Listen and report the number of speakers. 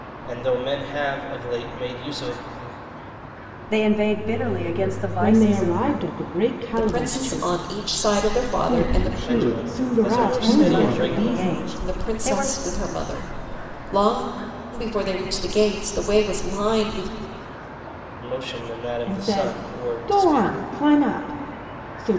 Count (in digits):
5